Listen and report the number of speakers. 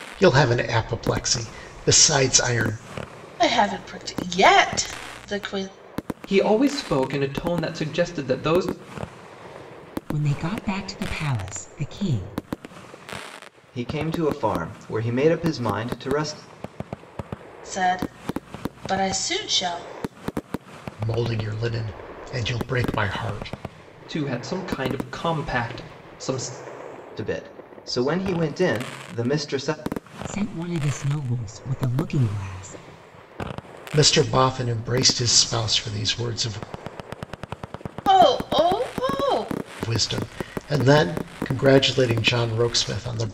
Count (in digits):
5